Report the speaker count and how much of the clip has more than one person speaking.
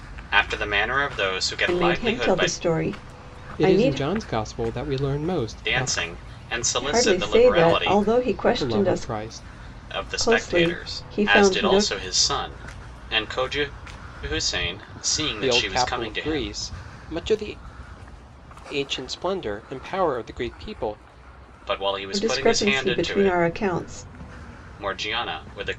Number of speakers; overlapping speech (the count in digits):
3, about 30%